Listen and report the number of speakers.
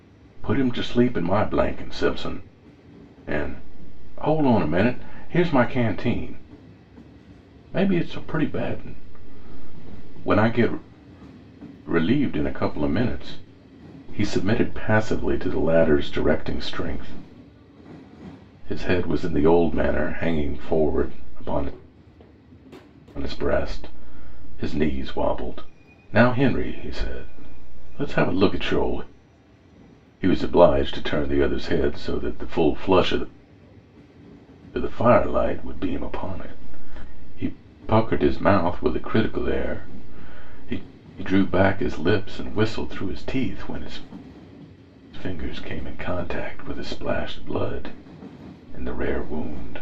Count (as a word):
one